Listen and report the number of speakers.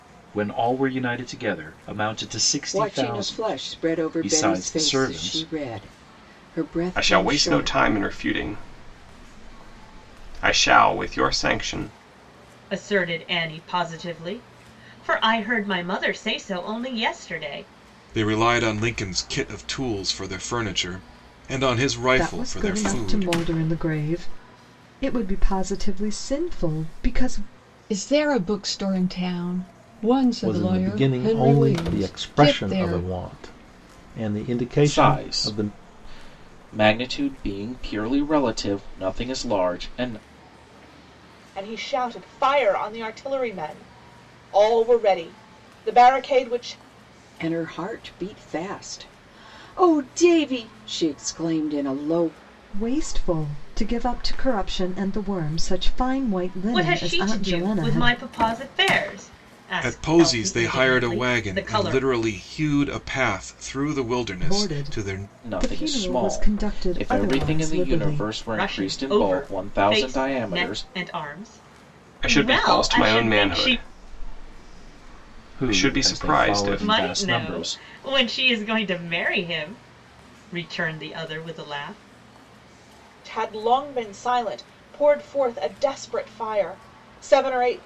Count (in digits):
10